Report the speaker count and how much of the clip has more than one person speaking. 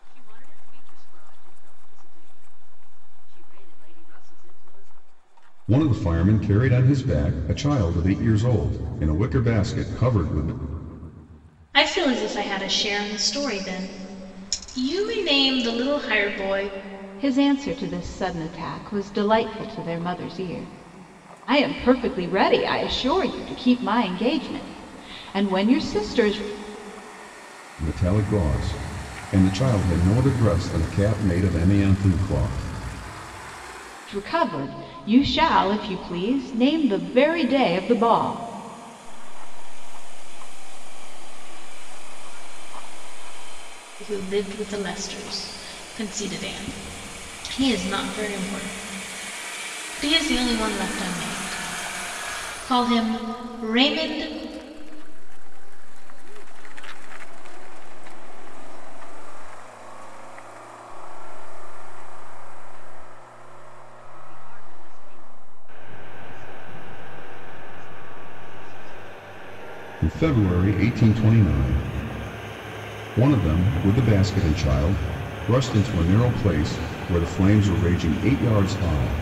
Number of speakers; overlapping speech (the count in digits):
4, no overlap